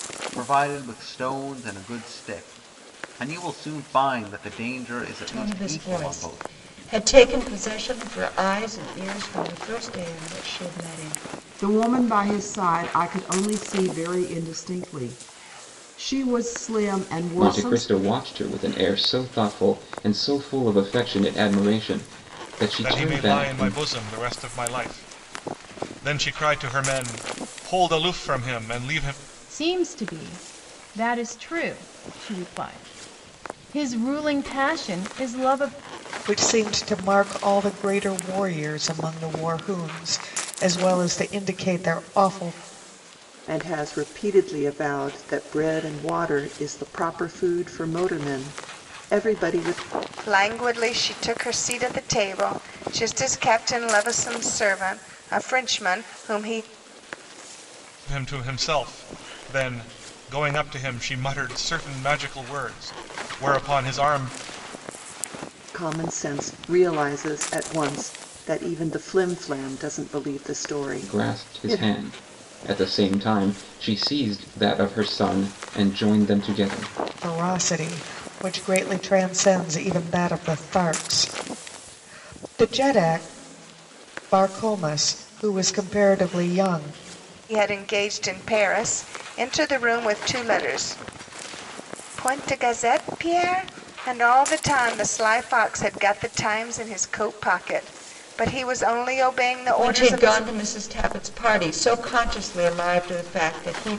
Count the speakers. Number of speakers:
9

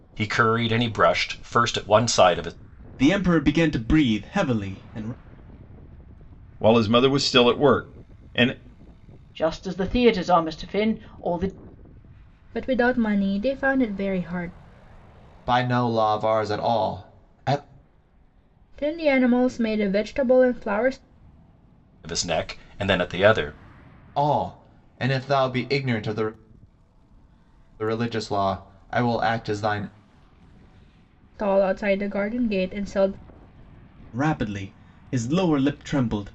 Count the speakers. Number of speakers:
6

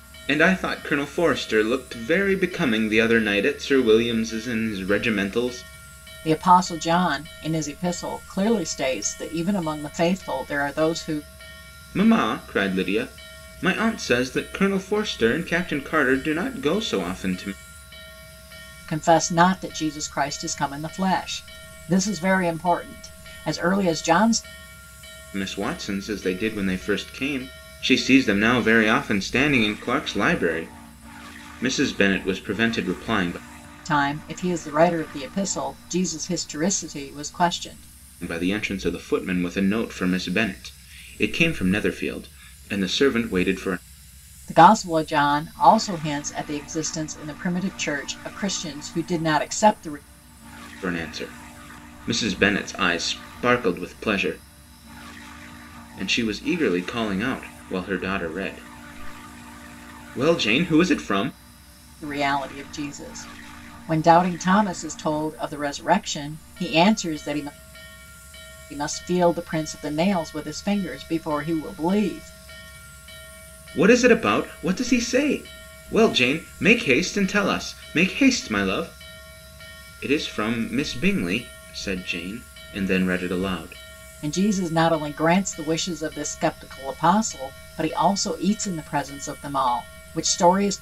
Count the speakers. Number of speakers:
2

